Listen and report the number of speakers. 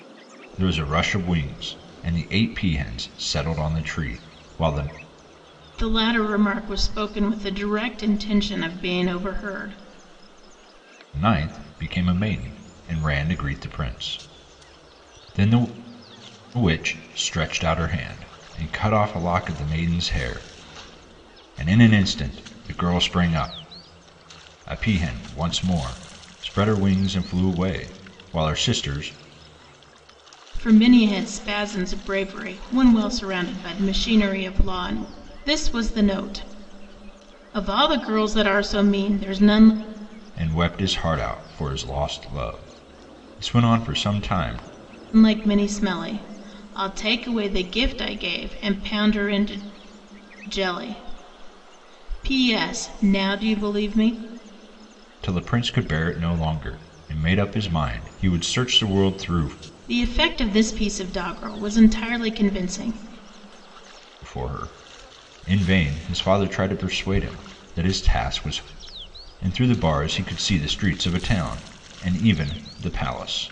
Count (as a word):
two